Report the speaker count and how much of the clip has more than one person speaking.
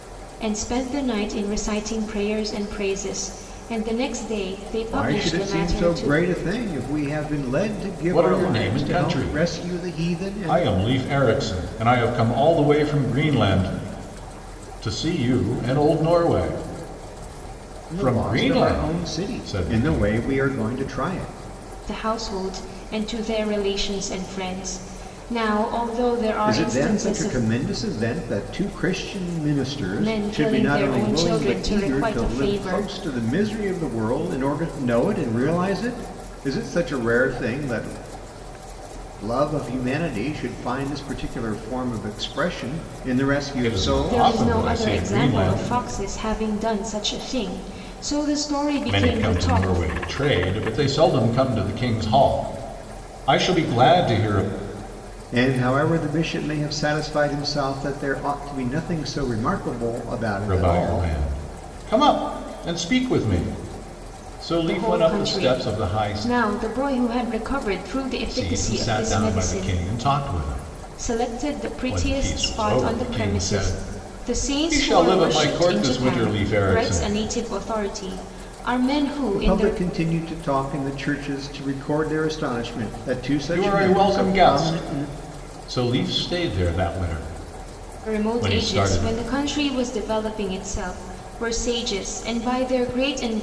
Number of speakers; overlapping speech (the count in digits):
3, about 27%